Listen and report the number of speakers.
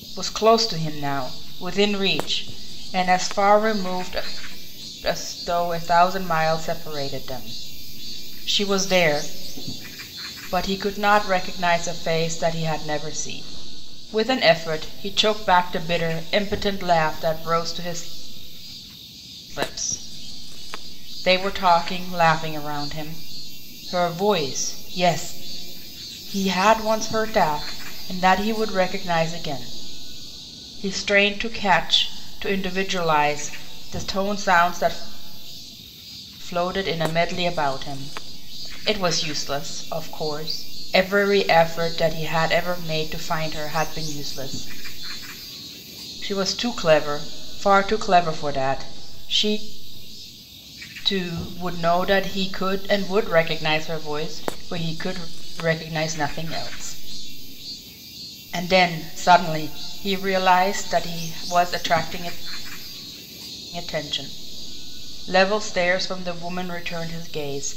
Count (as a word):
one